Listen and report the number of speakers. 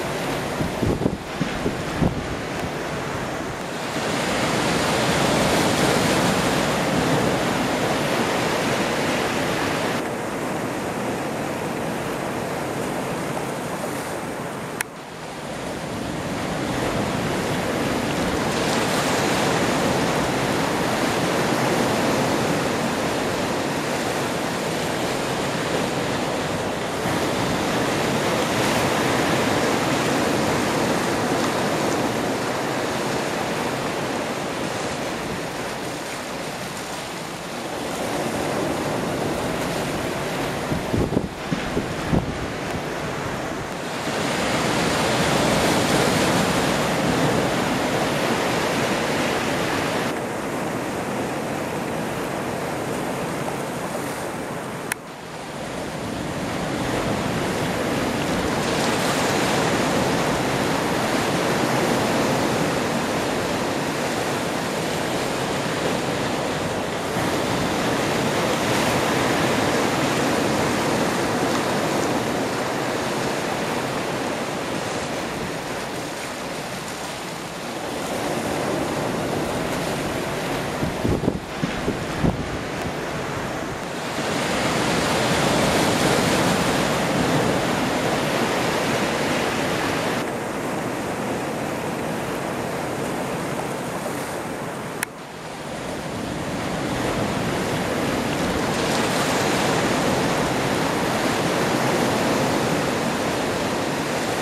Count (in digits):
0